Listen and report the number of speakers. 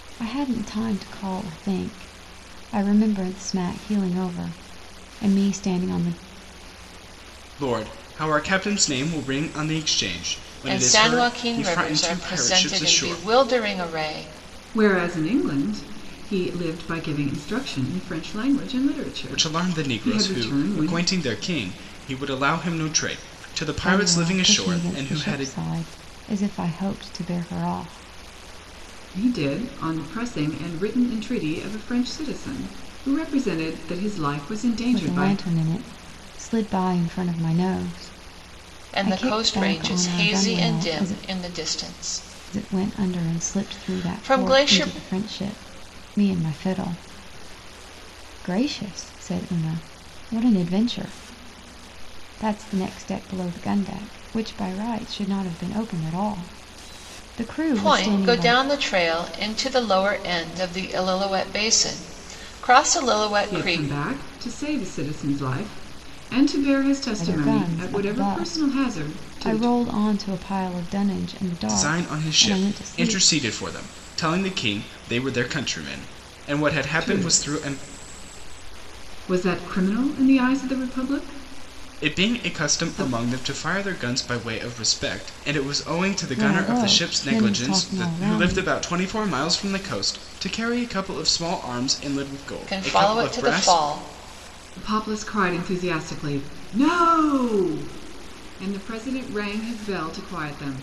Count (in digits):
4